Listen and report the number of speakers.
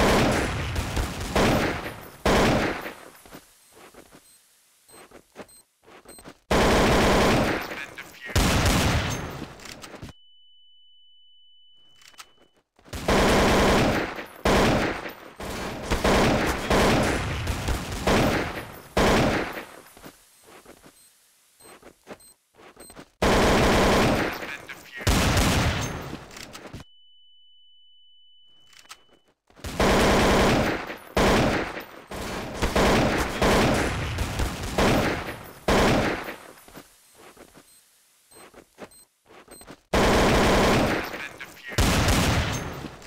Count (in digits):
0